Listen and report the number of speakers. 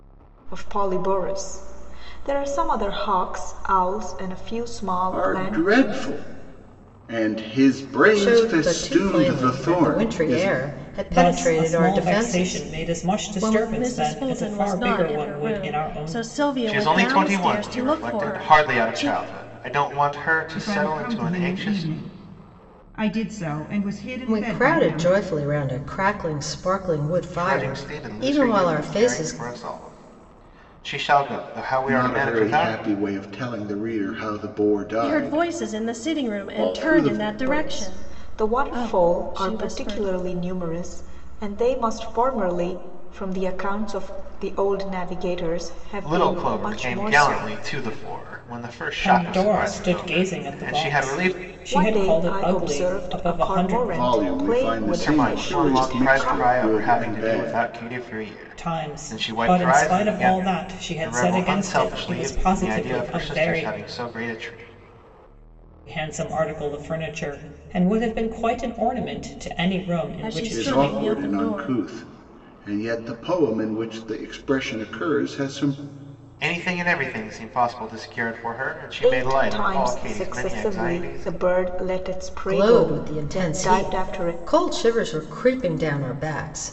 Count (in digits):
7